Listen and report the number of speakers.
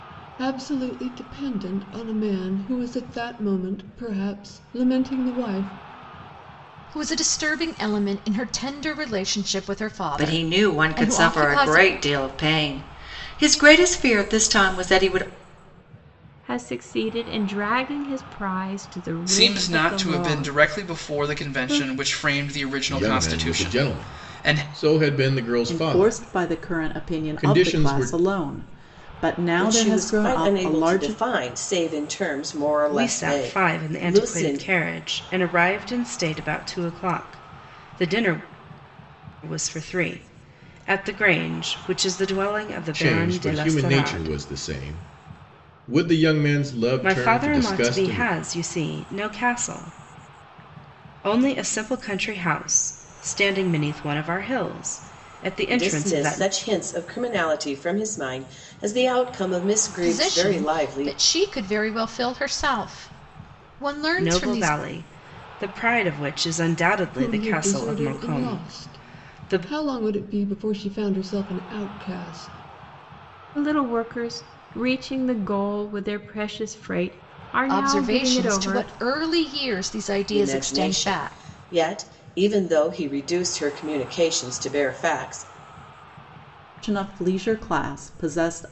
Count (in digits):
9